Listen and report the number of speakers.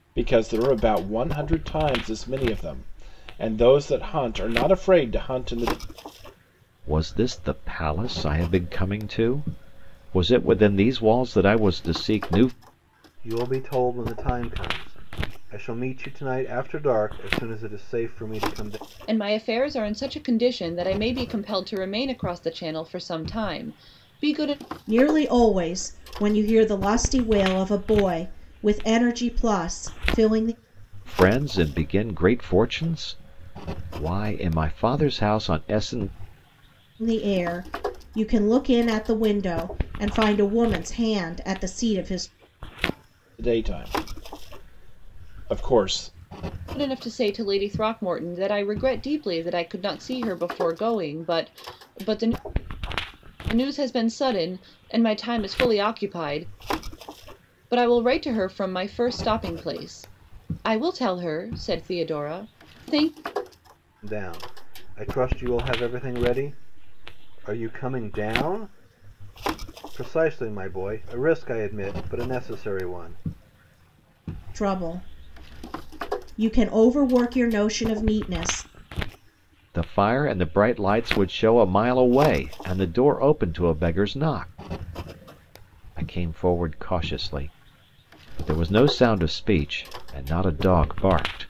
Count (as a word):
five